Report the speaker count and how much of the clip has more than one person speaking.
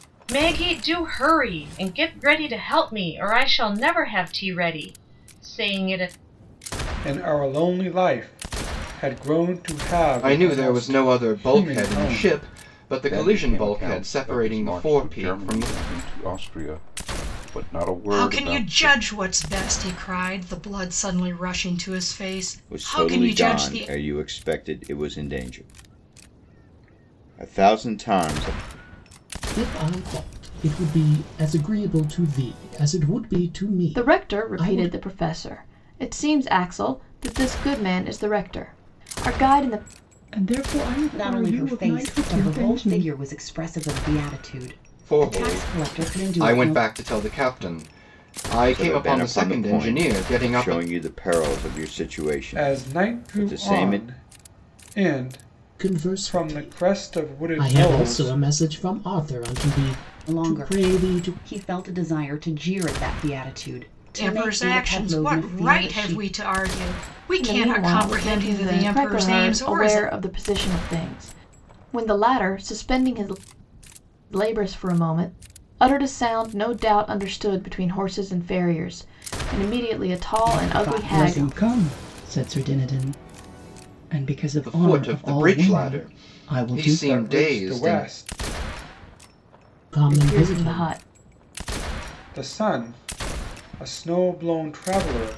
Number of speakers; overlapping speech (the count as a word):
ten, about 31%